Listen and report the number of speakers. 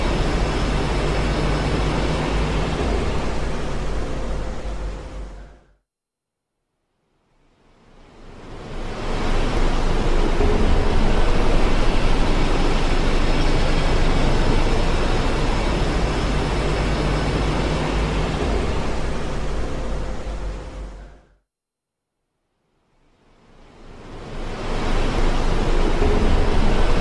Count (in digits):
0